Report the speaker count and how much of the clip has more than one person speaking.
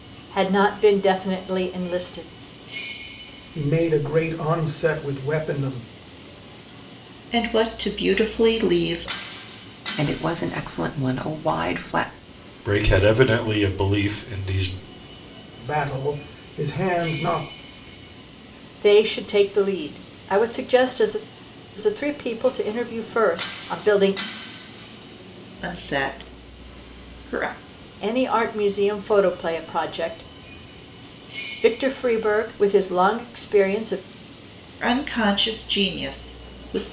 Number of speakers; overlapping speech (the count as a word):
five, no overlap